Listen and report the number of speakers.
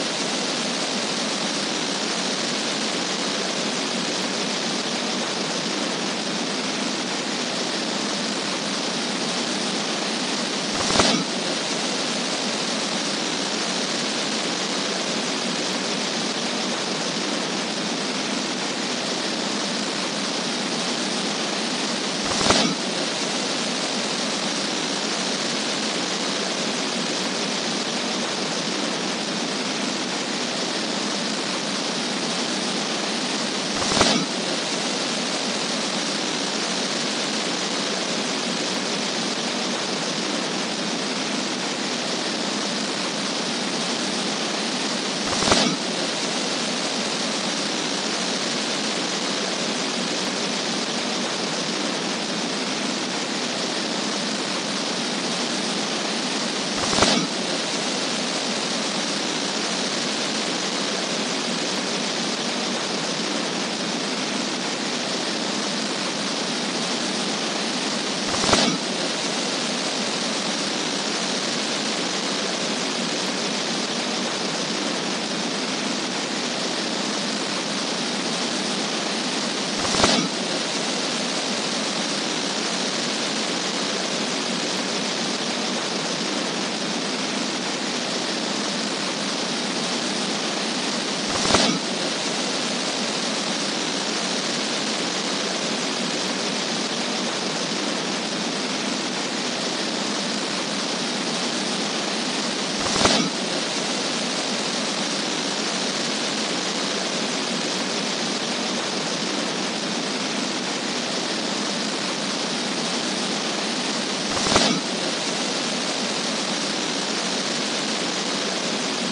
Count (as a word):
zero